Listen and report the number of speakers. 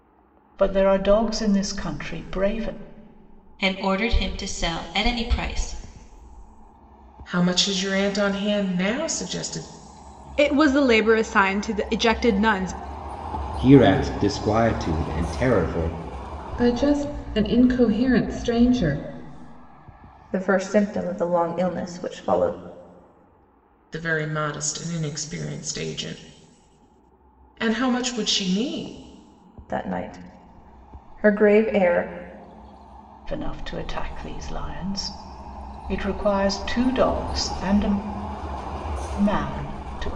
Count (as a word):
seven